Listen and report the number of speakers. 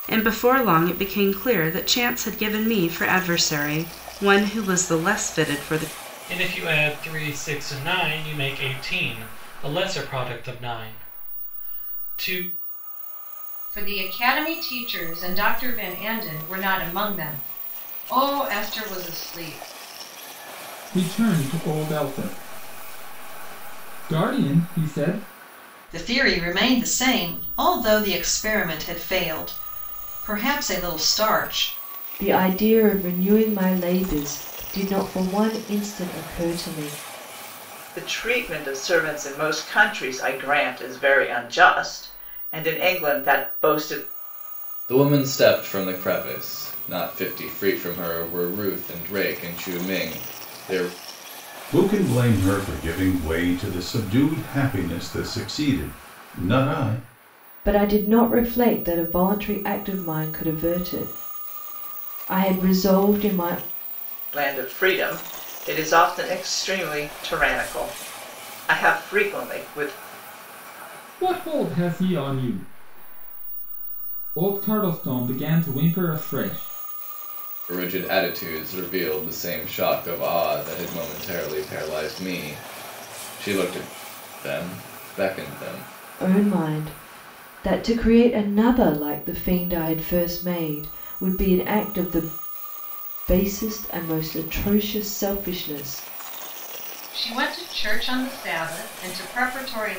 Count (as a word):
nine